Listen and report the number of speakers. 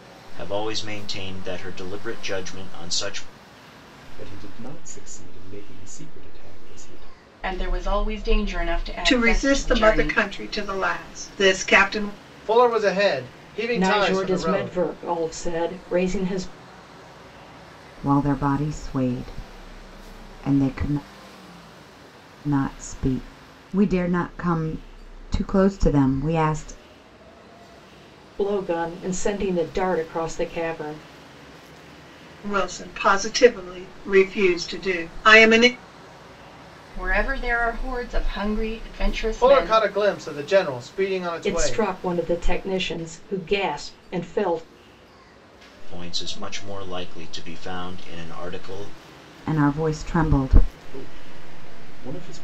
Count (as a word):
seven